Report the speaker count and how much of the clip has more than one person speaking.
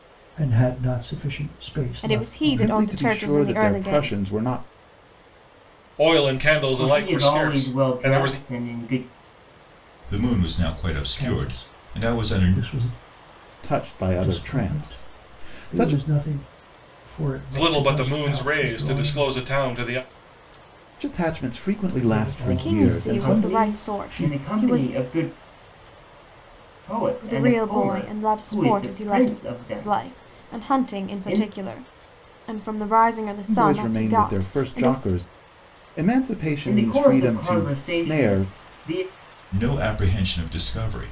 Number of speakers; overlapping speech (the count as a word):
six, about 47%